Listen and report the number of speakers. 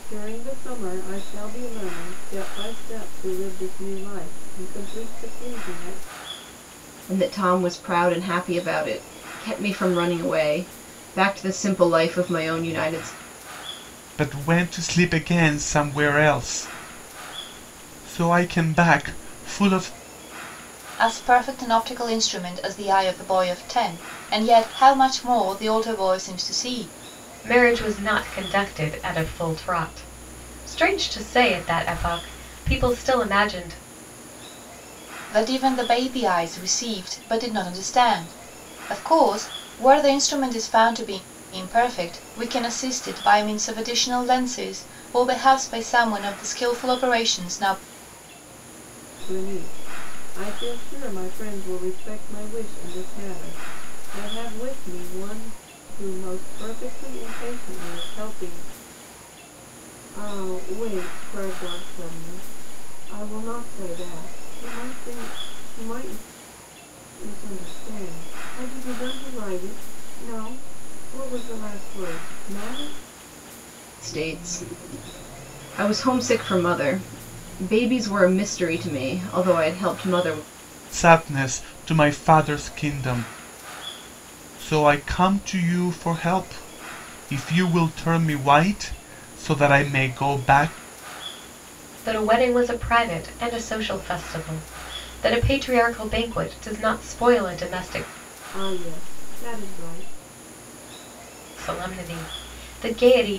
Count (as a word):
five